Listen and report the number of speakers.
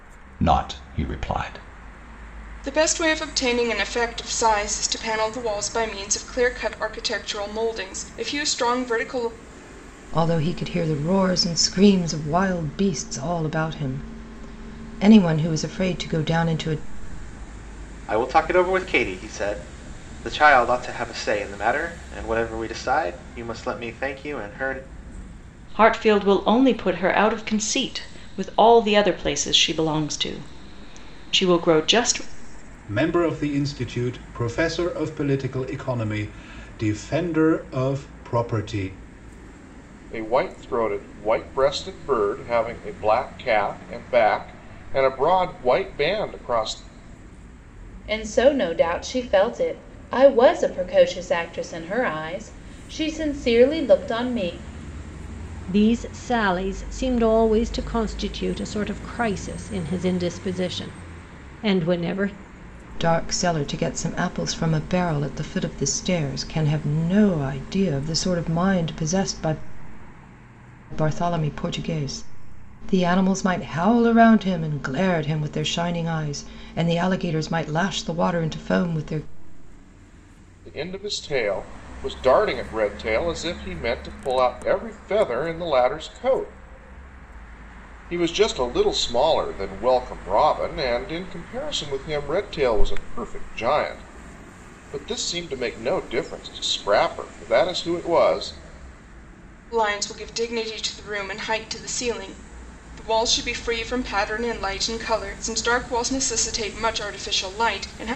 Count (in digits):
9